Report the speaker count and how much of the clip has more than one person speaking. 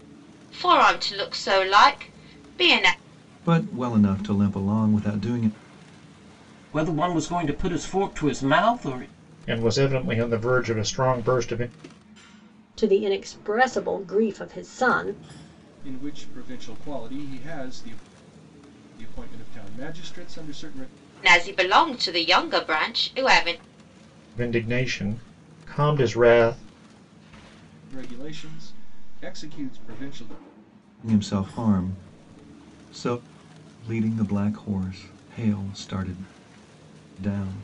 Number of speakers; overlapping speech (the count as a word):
six, no overlap